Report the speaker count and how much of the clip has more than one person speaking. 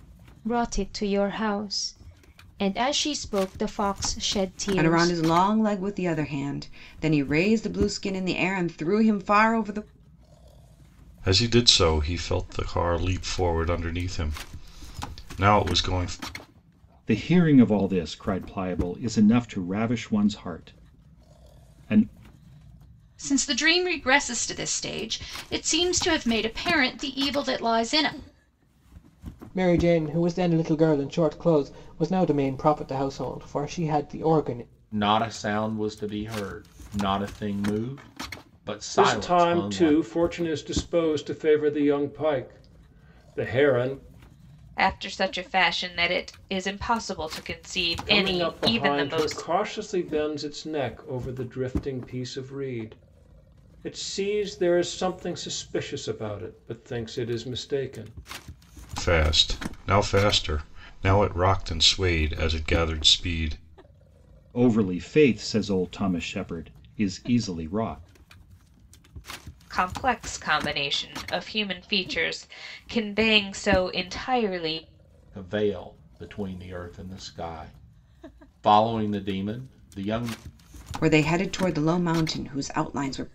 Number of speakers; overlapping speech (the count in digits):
9, about 4%